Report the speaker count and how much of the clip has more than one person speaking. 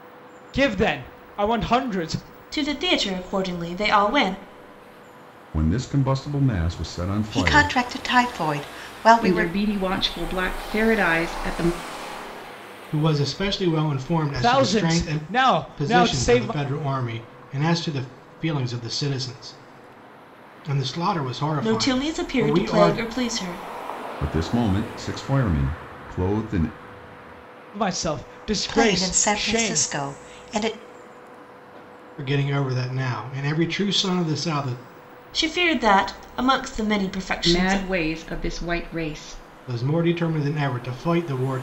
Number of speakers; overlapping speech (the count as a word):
six, about 14%